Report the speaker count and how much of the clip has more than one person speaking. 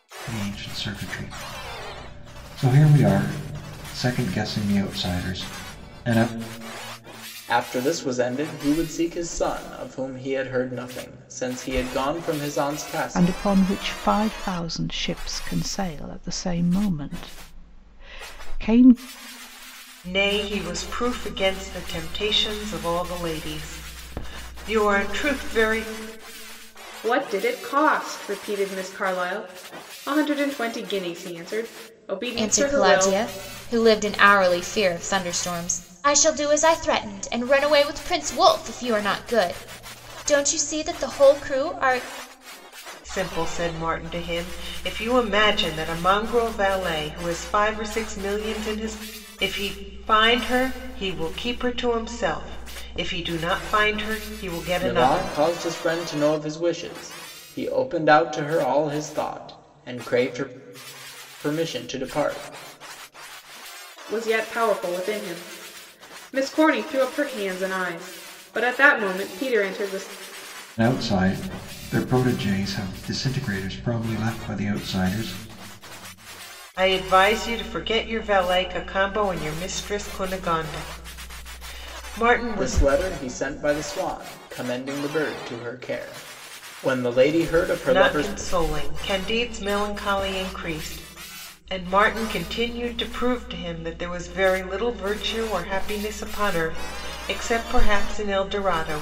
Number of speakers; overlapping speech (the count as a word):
six, about 3%